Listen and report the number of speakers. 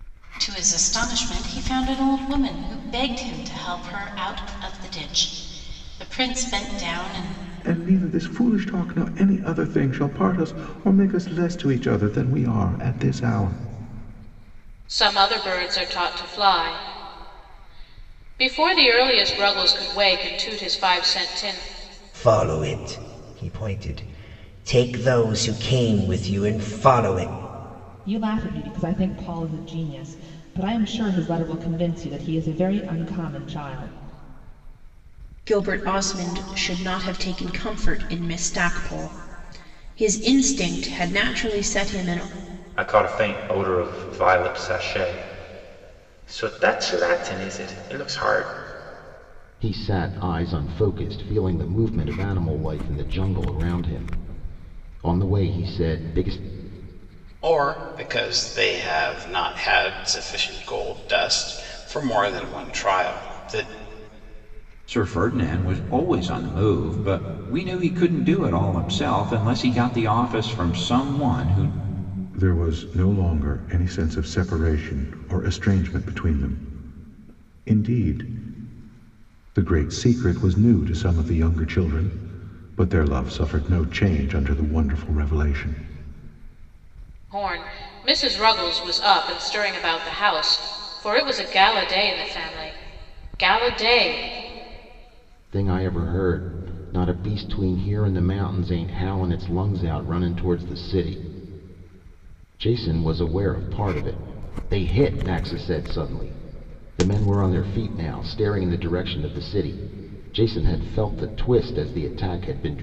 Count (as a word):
ten